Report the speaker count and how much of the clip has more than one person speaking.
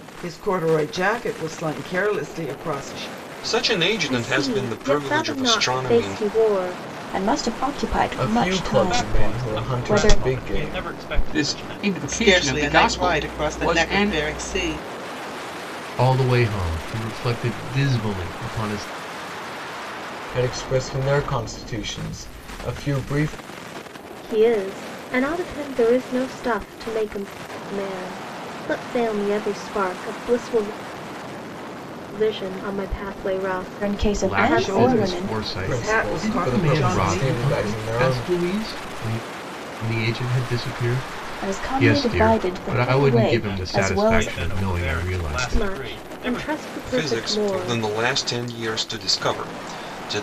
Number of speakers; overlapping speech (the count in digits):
9, about 36%